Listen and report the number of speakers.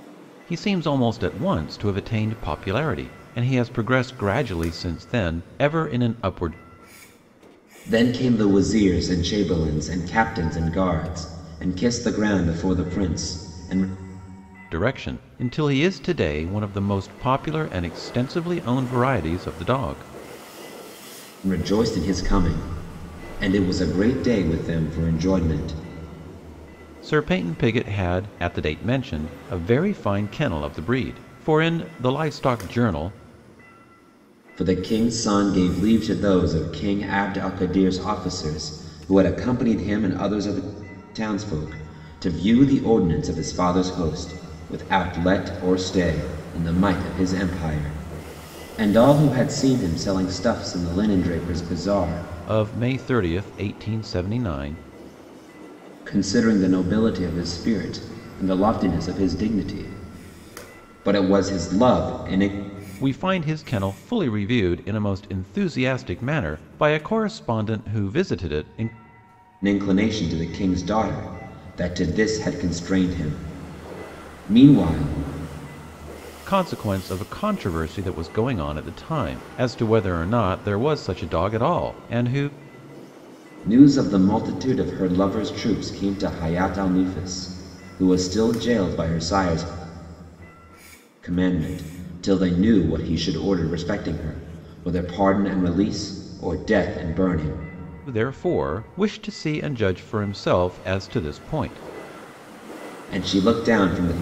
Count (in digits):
2